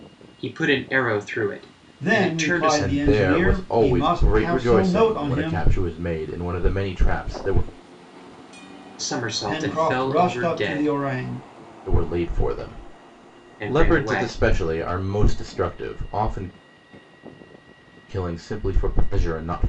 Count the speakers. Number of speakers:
three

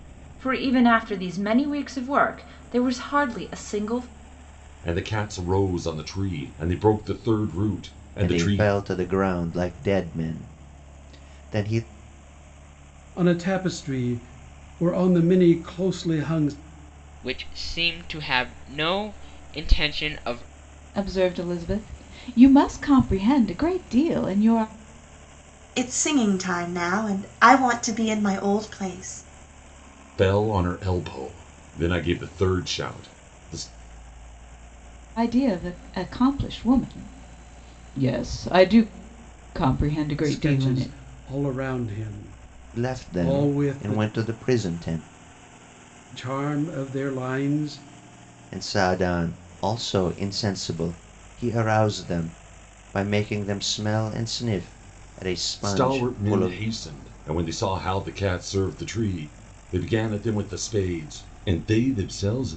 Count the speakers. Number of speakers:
seven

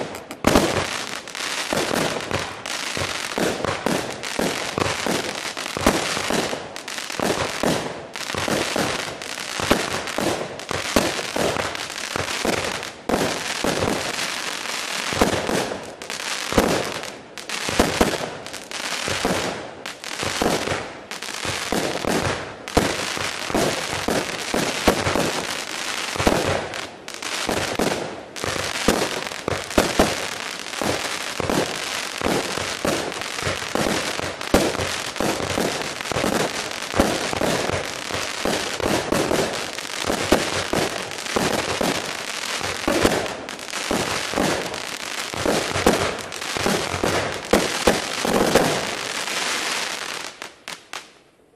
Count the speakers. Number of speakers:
zero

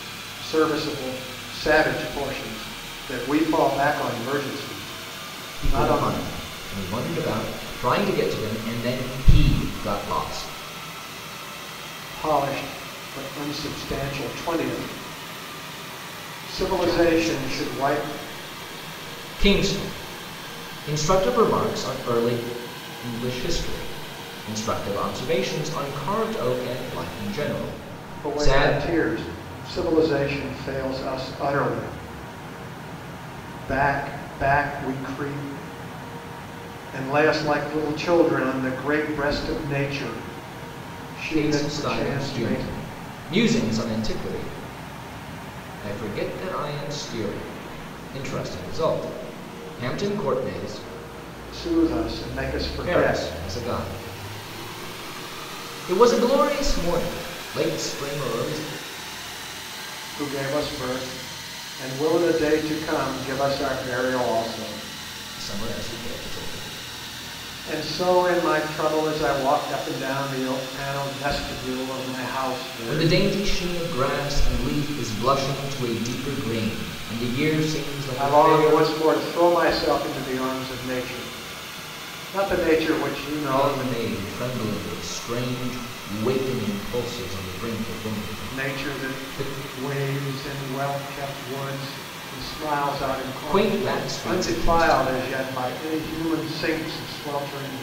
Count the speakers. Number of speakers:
two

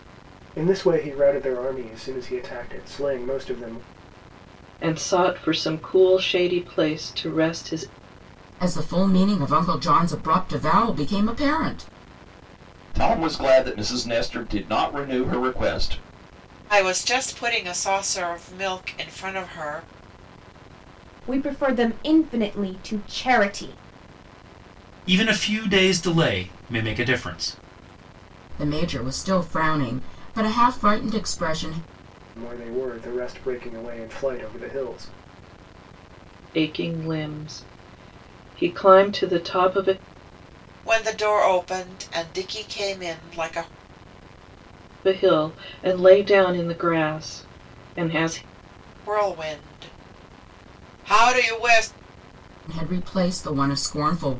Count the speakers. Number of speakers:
seven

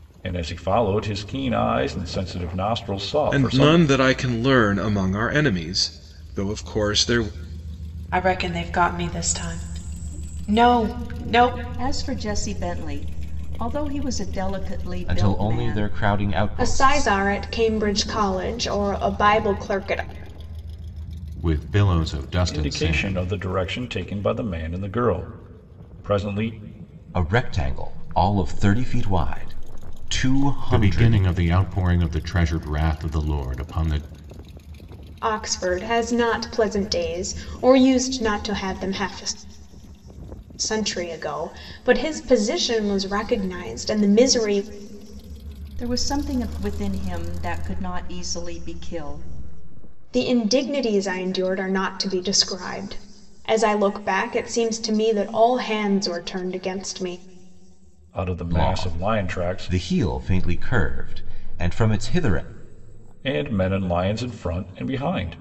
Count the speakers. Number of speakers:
seven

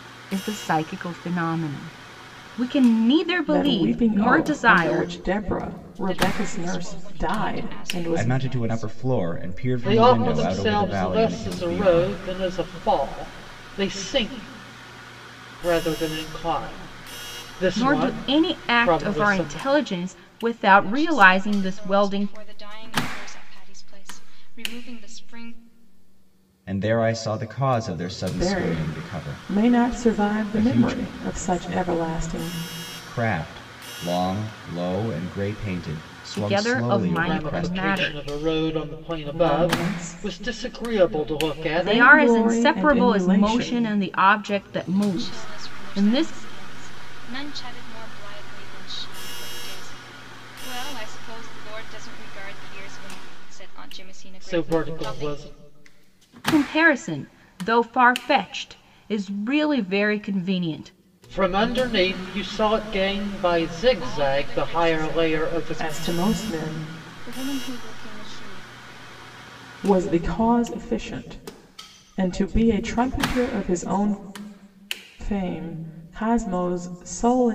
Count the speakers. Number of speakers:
five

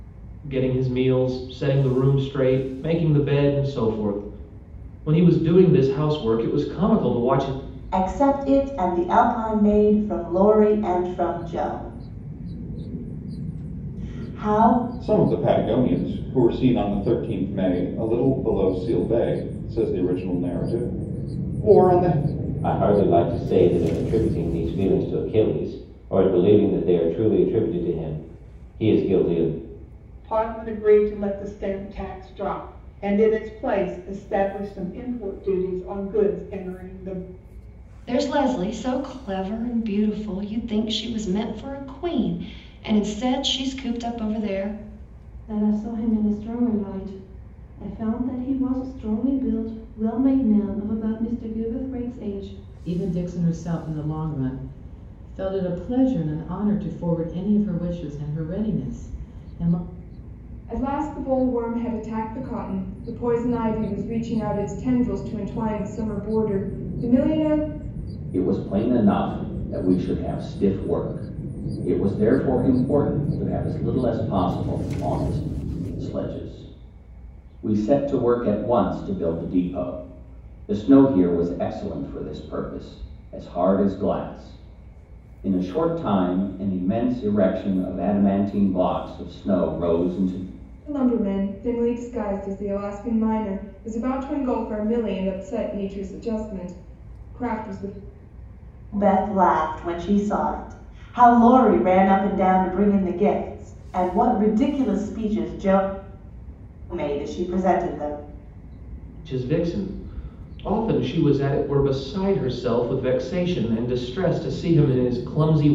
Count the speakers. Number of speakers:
ten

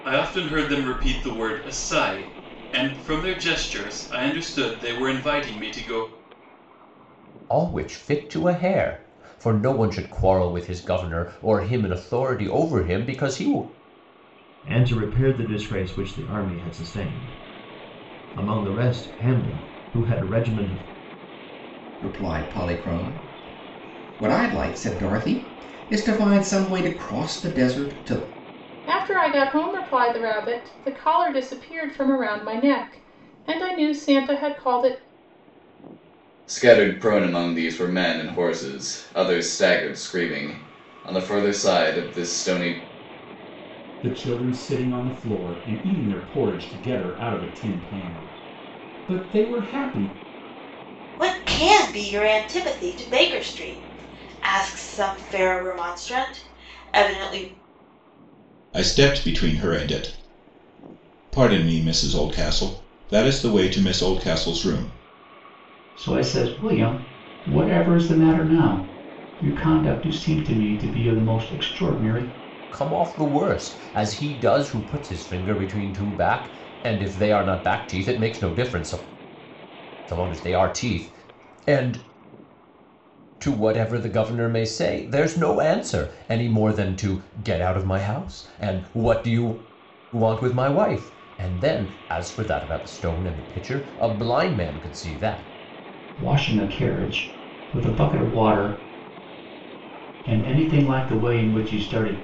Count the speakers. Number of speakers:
ten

